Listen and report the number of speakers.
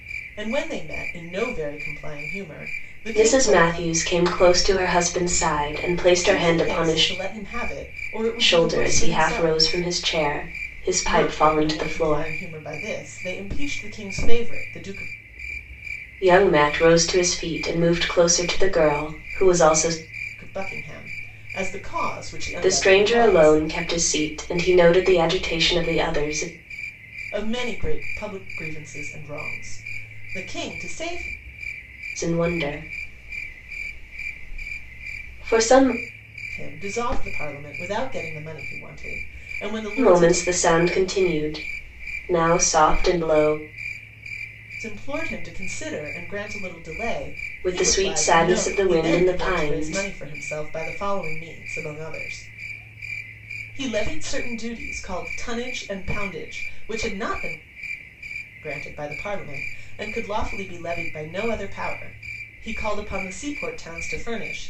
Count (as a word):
two